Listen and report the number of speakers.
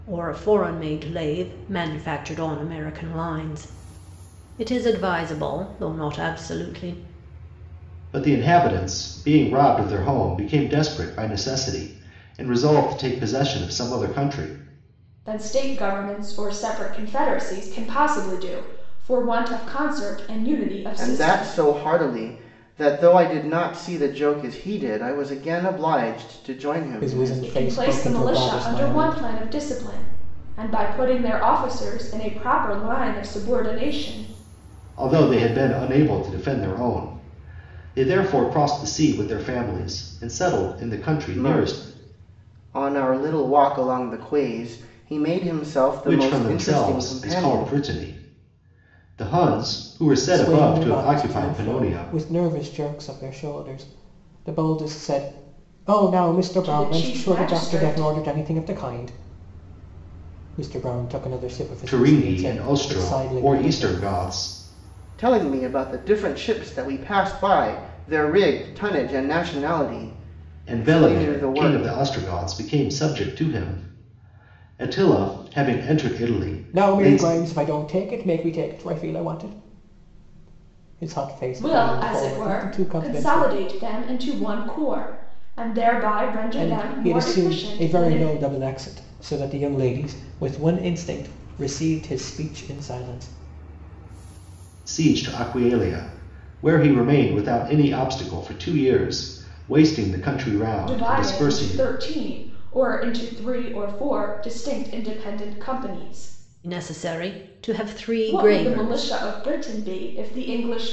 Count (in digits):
5